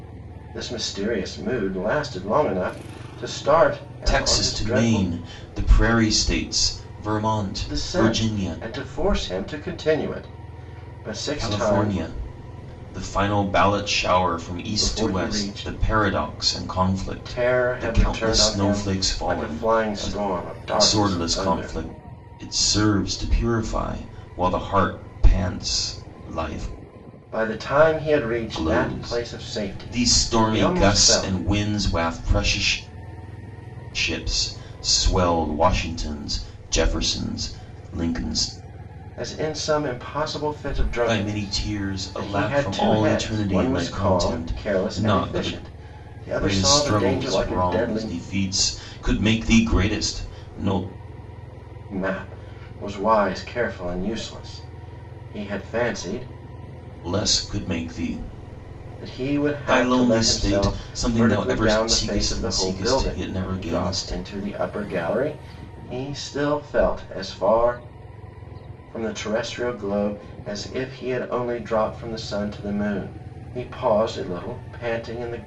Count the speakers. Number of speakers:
two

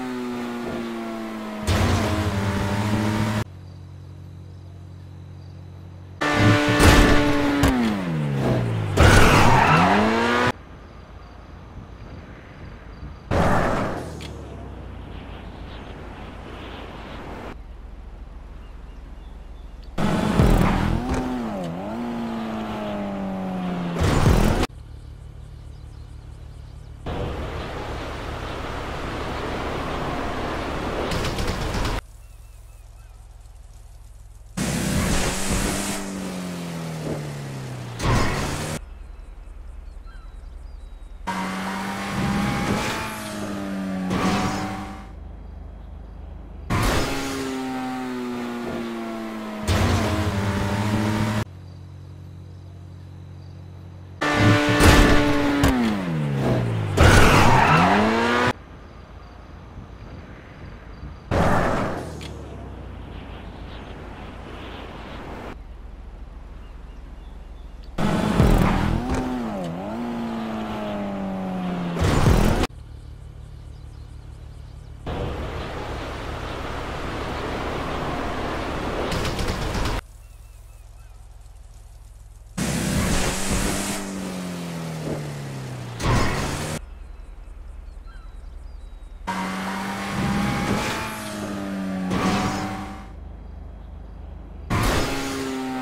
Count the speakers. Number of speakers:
zero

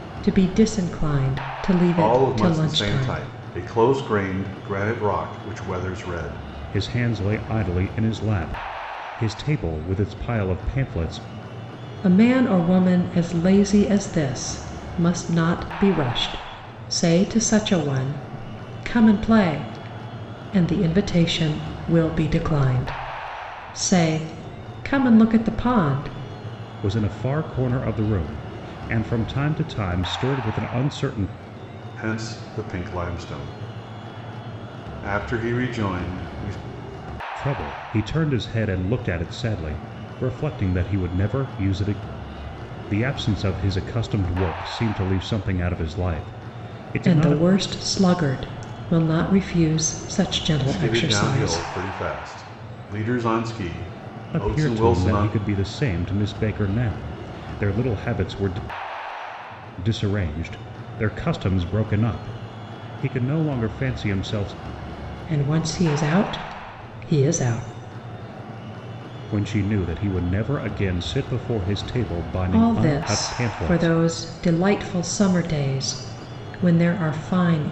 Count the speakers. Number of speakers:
three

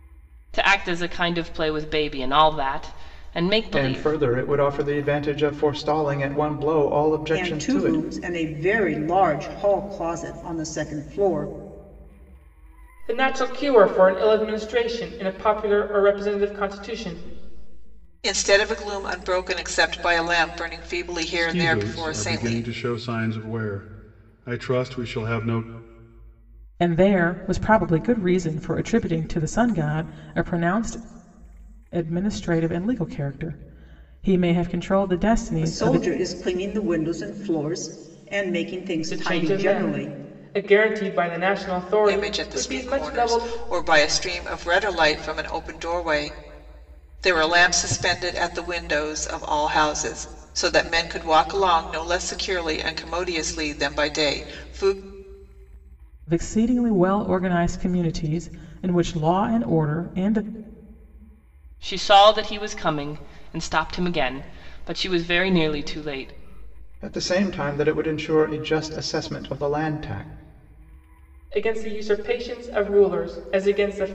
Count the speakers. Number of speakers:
seven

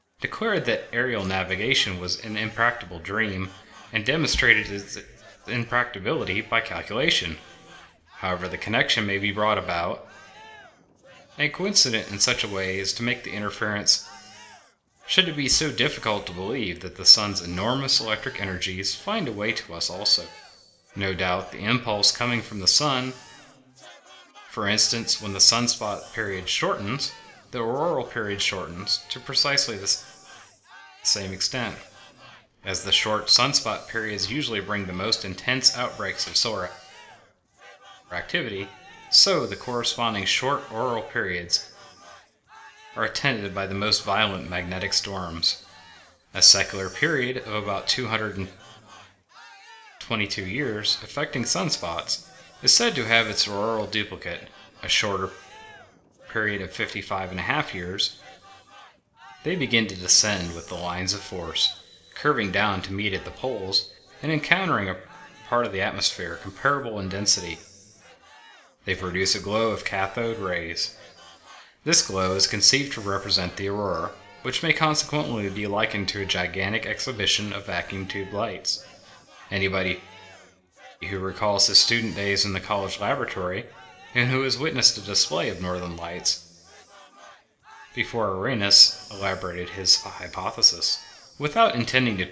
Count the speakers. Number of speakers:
one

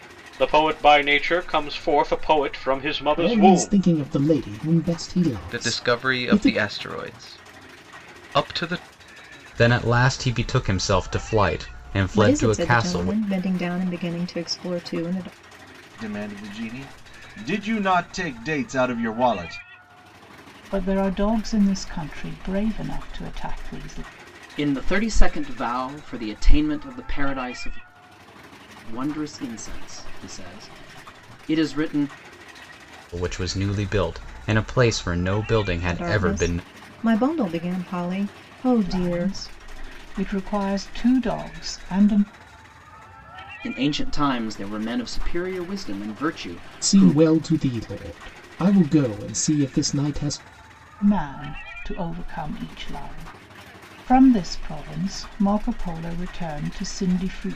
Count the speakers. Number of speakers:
eight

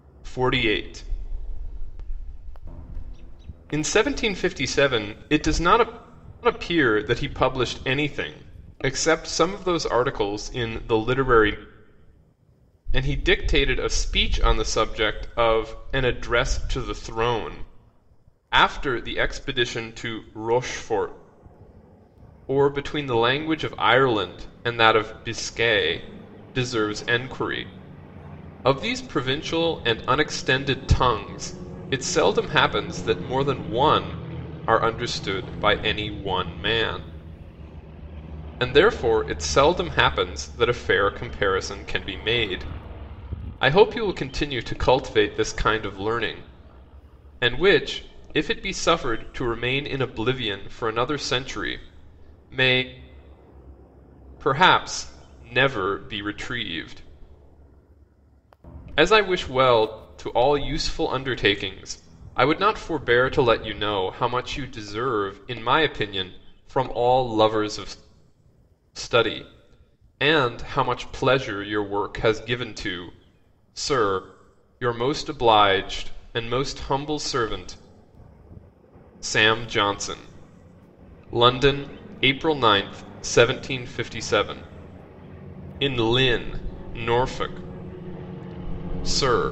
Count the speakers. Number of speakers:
one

